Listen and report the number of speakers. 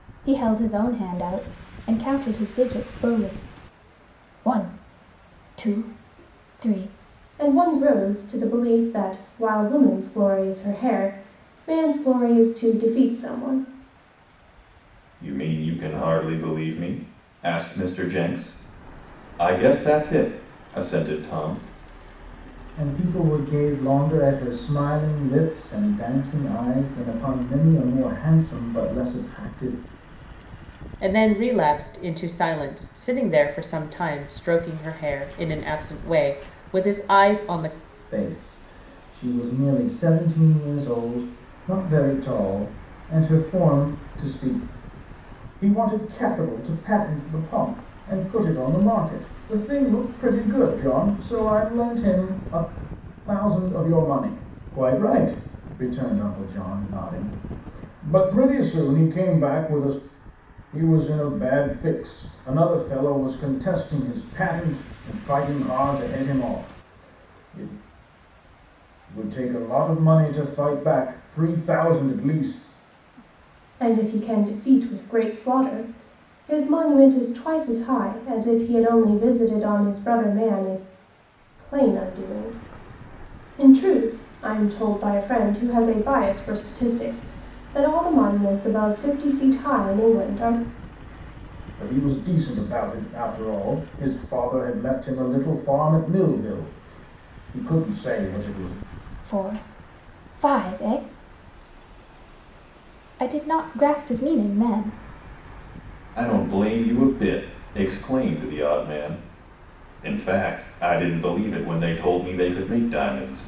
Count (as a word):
five